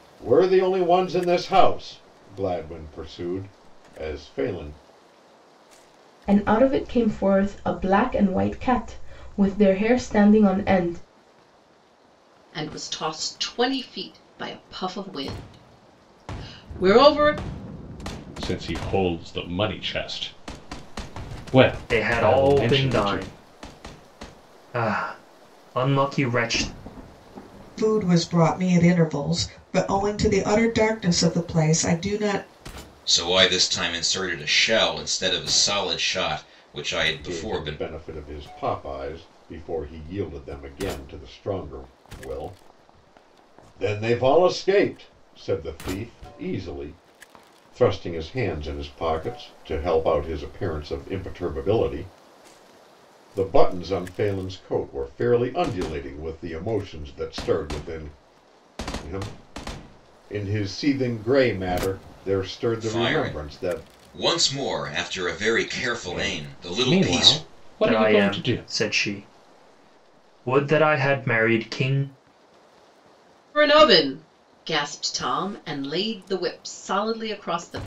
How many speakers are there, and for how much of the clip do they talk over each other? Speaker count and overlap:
7, about 7%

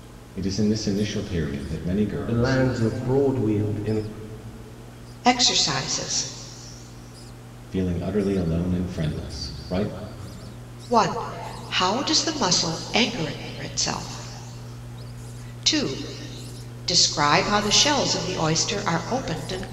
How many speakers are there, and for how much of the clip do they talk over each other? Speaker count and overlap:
3, about 2%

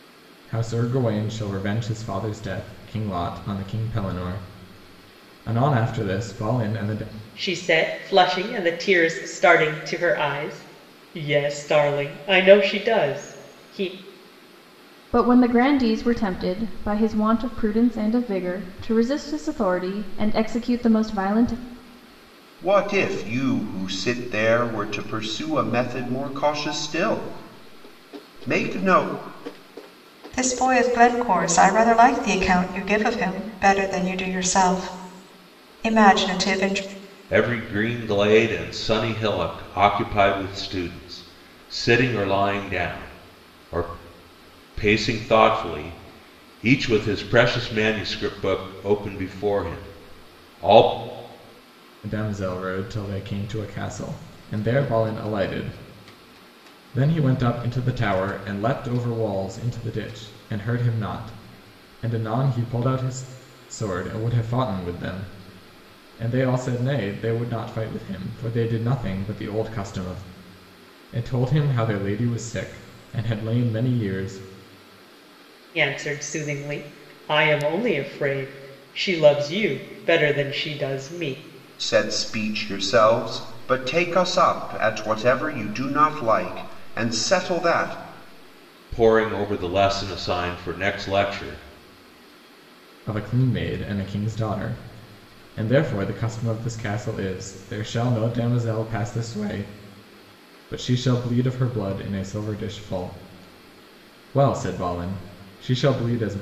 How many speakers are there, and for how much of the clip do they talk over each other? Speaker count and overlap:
6, no overlap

